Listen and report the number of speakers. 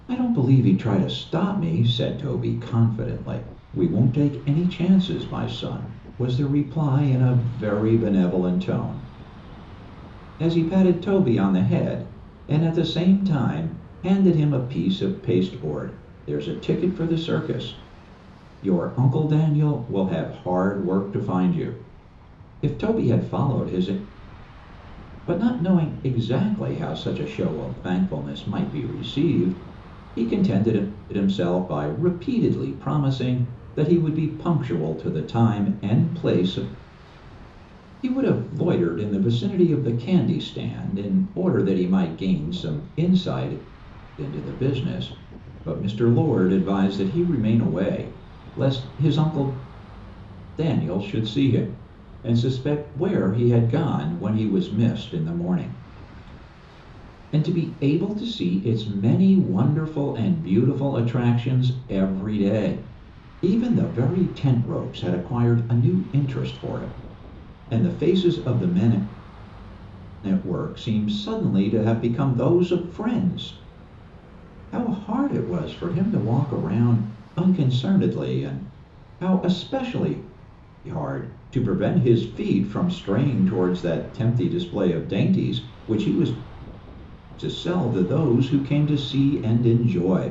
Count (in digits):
1